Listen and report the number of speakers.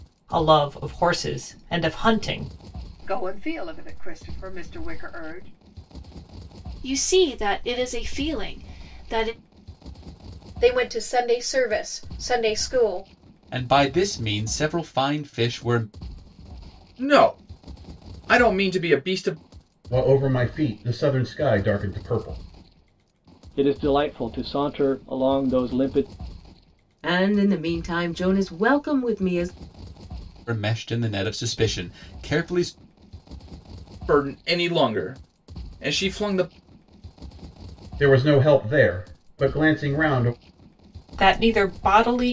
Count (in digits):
9